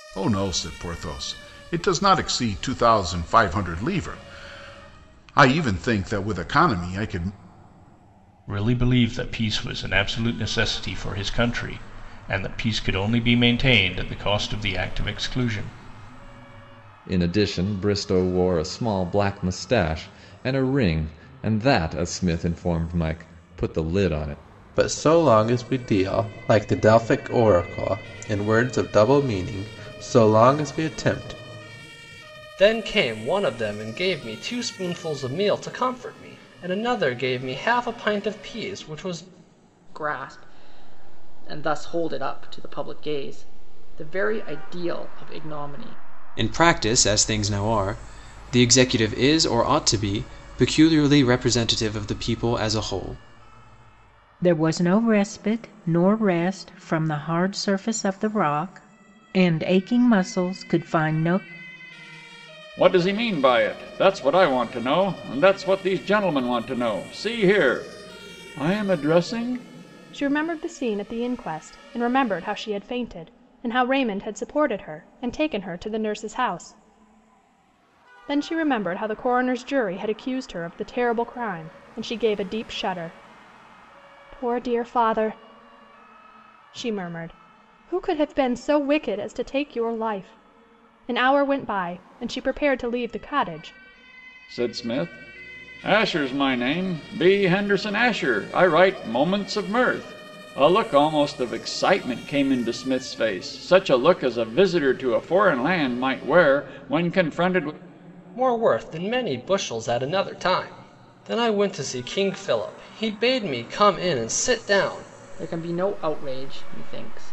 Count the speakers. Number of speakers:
10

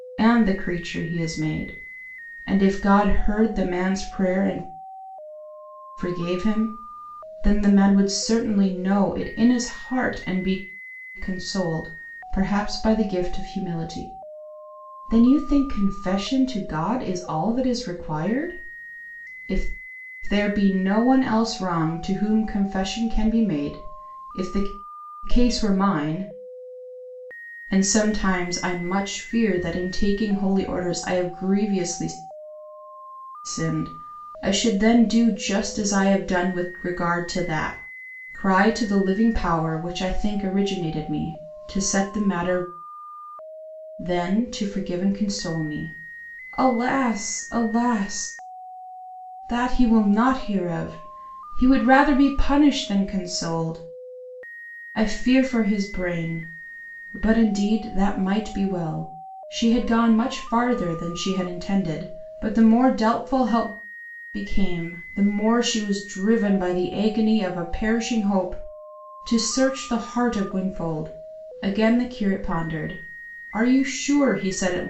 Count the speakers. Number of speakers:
1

